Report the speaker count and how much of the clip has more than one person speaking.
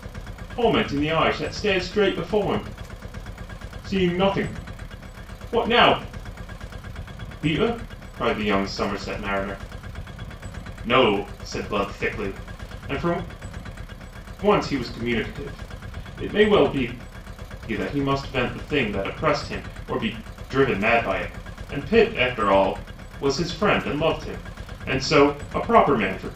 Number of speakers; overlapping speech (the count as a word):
one, no overlap